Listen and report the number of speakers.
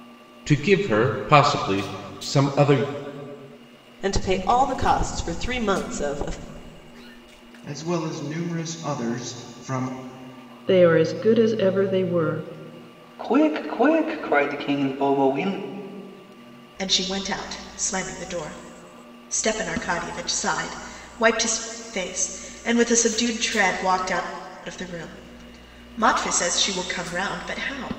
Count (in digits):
6